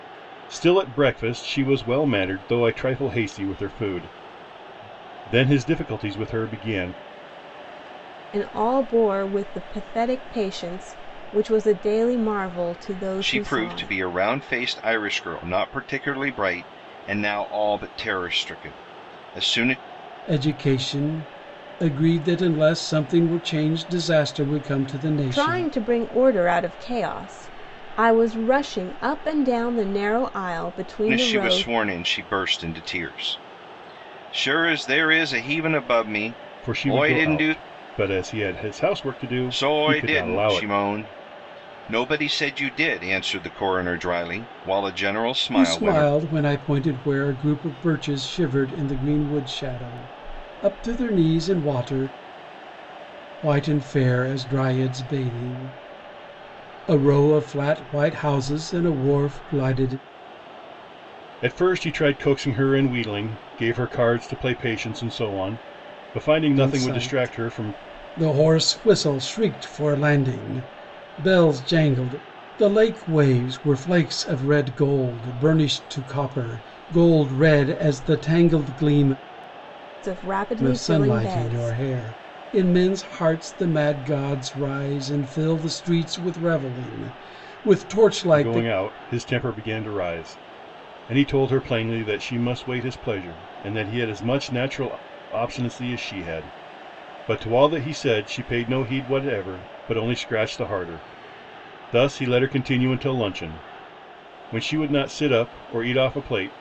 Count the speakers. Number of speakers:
four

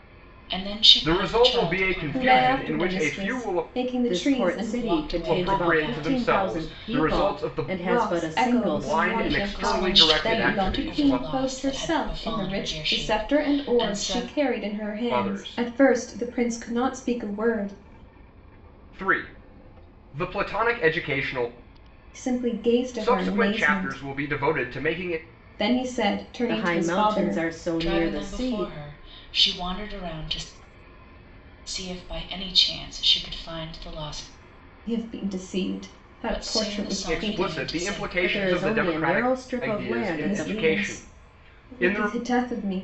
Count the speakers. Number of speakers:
four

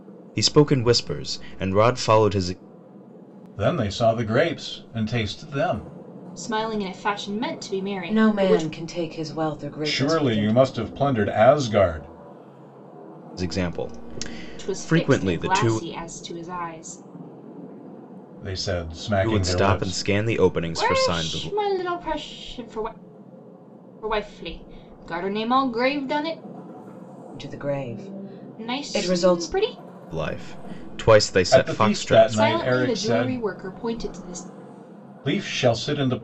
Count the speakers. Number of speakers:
four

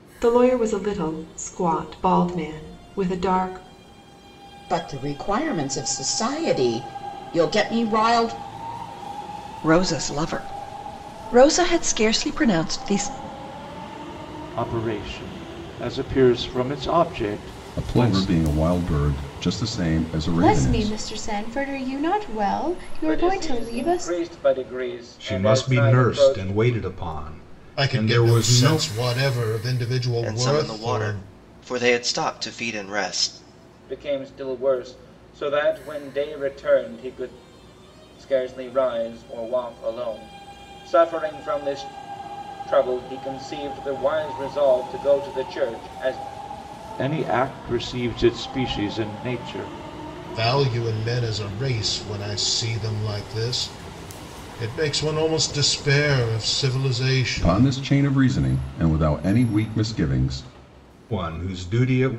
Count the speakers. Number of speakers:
ten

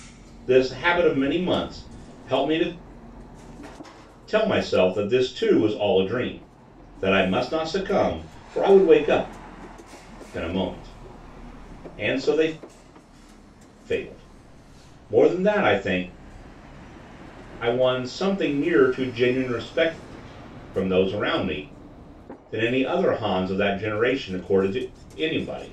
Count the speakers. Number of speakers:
one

